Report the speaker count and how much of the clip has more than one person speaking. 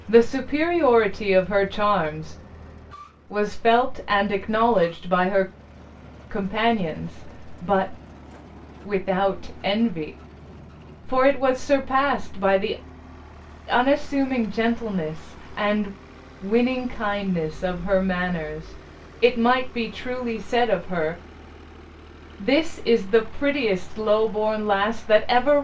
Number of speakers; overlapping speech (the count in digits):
1, no overlap